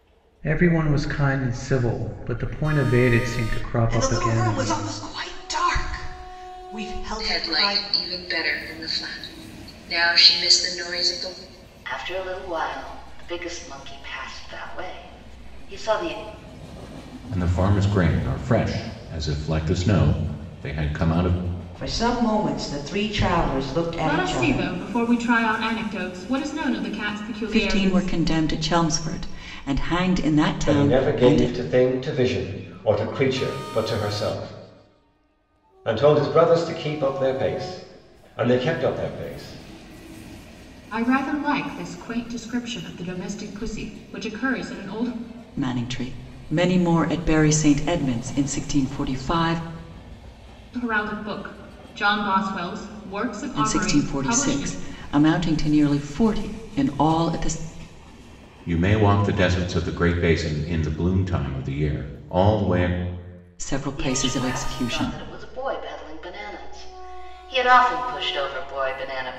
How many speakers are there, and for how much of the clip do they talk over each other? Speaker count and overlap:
nine, about 9%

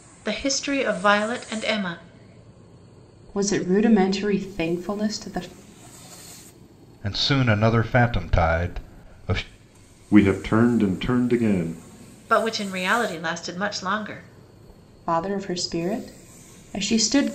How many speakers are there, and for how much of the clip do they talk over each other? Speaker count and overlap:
four, no overlap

